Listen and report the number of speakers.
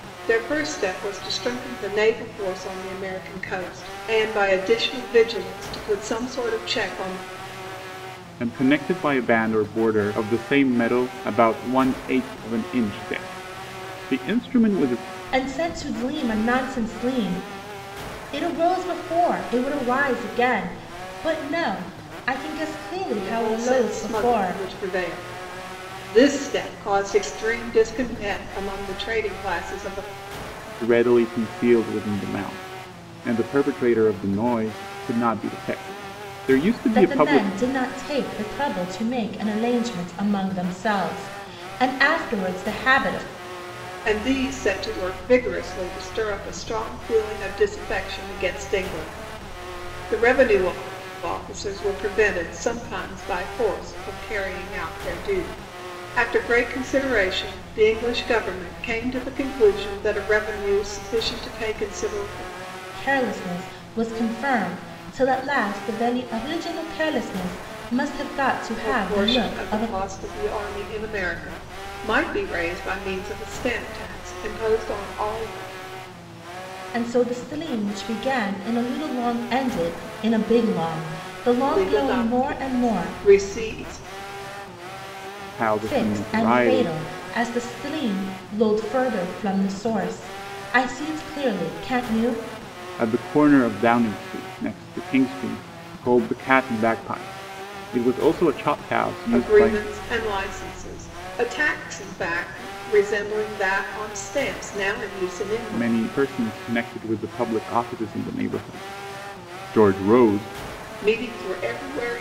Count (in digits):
3